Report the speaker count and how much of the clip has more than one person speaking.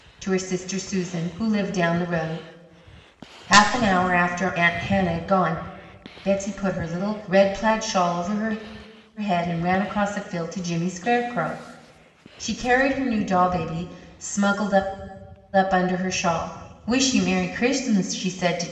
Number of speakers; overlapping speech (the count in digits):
1, no overlap